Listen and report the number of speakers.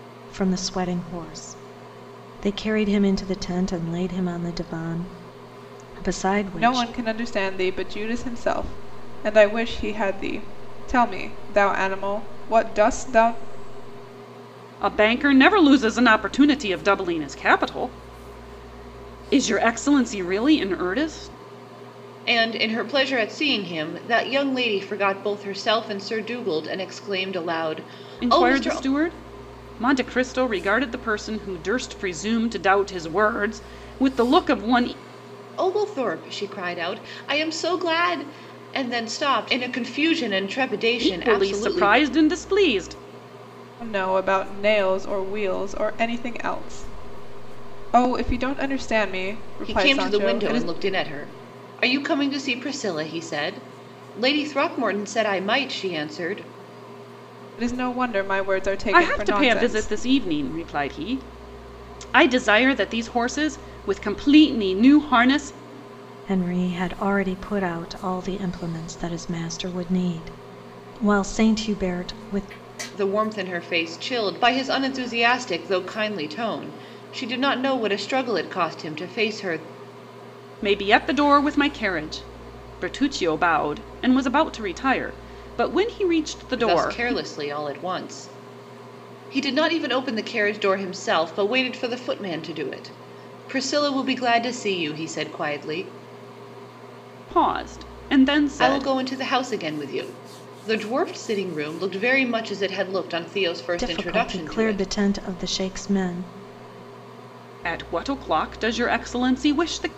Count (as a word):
four